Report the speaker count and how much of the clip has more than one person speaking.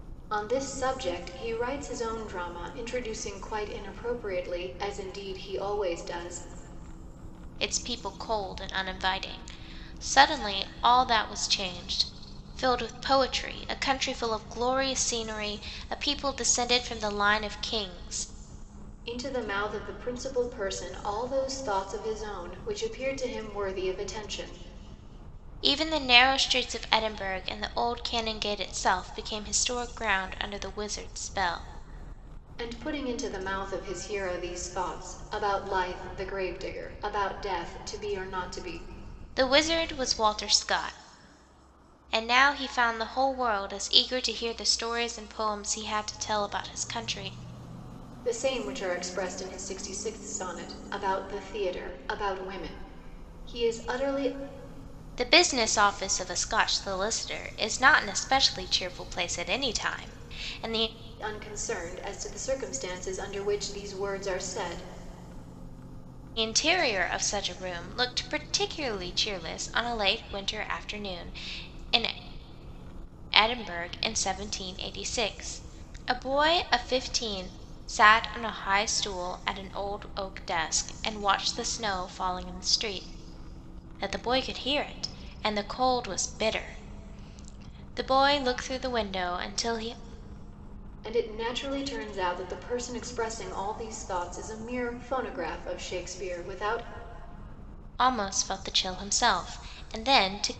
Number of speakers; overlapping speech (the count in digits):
2, no overlap